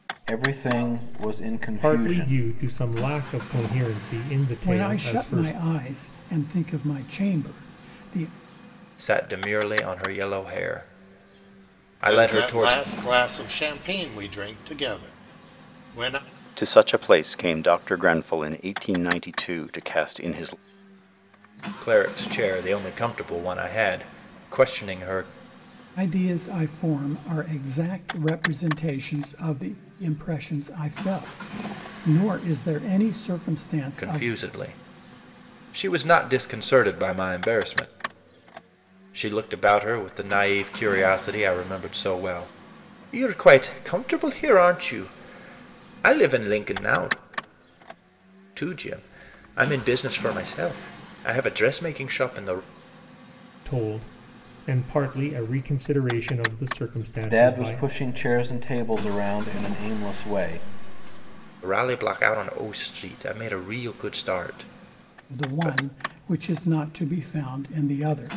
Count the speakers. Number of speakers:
six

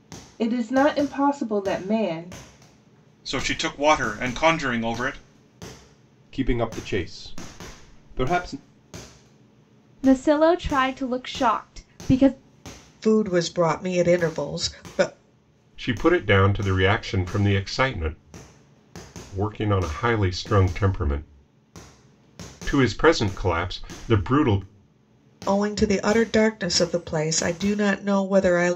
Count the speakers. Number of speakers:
six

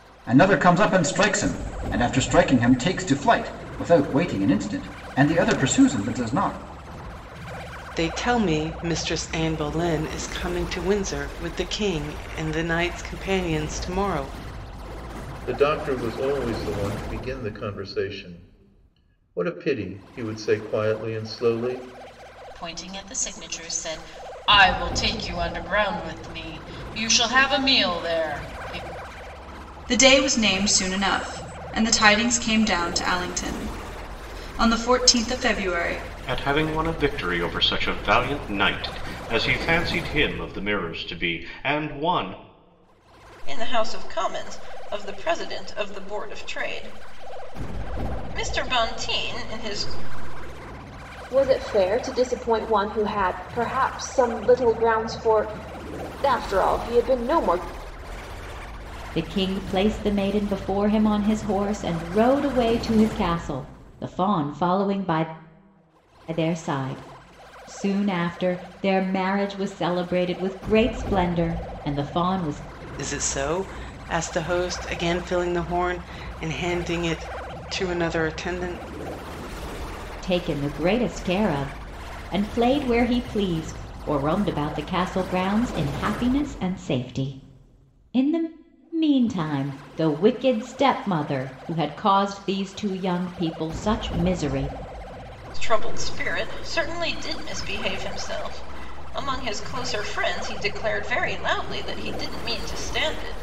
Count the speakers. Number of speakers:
nine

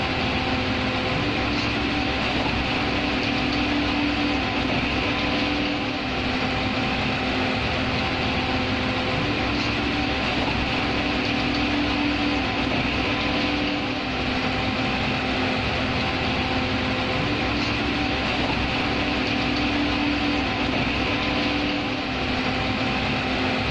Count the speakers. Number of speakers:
zero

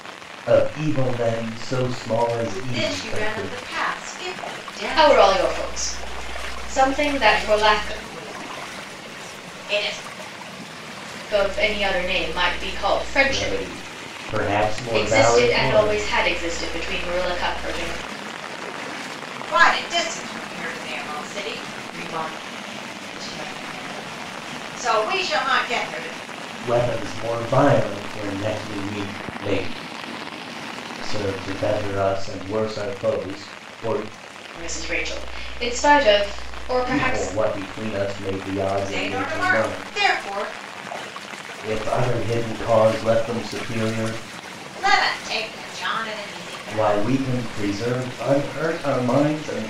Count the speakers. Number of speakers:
three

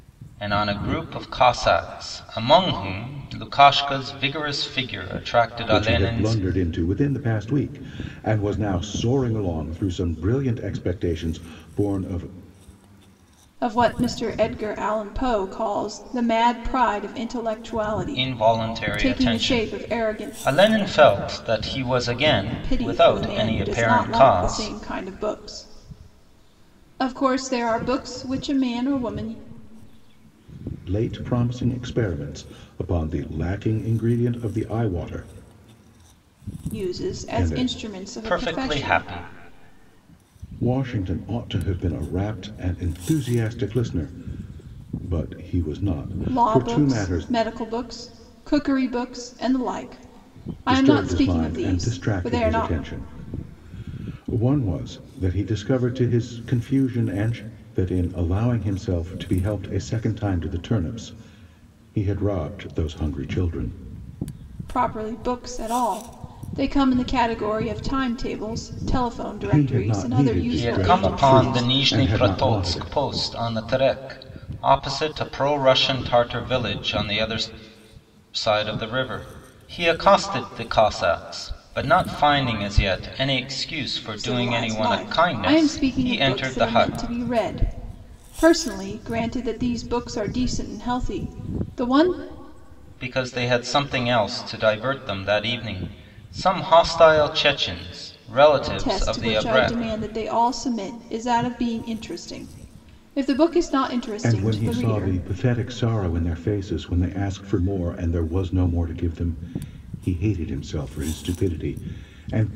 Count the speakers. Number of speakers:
three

